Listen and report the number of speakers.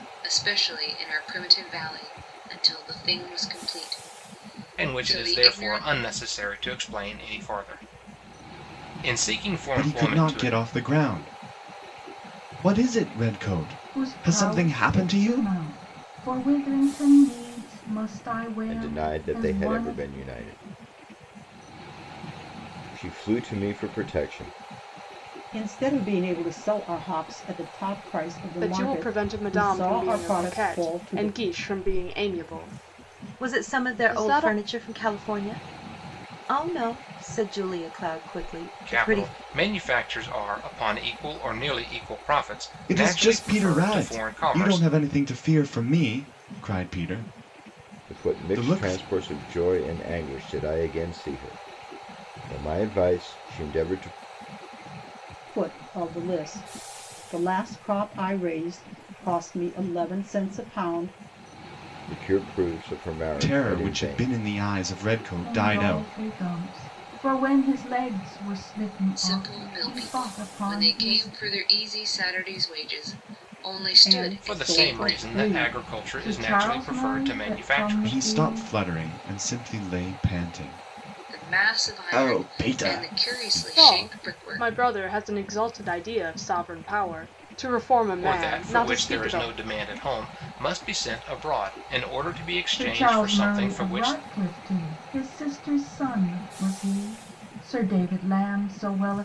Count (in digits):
8